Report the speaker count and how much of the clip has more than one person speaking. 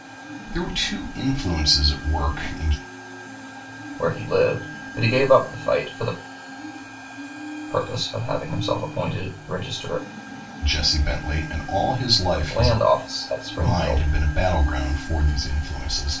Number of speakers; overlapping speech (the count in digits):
2, about 6%